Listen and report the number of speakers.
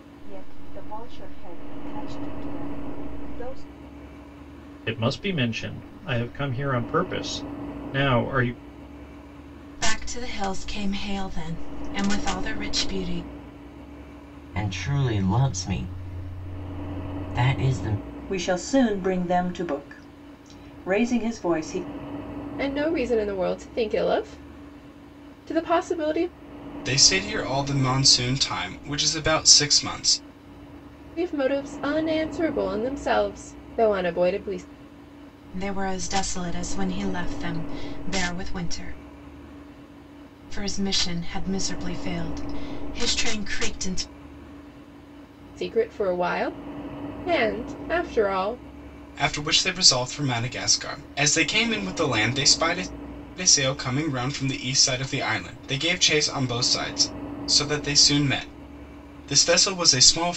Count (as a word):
seven